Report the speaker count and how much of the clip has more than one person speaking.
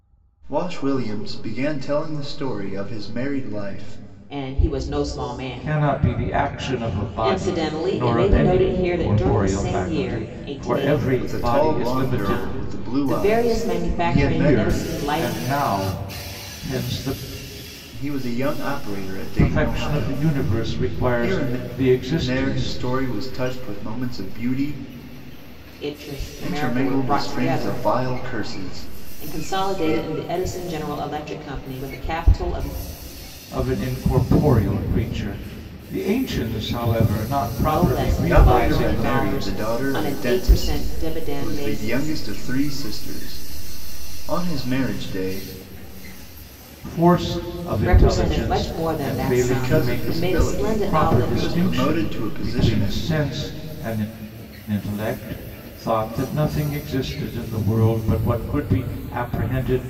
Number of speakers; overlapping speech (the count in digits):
3, about 41%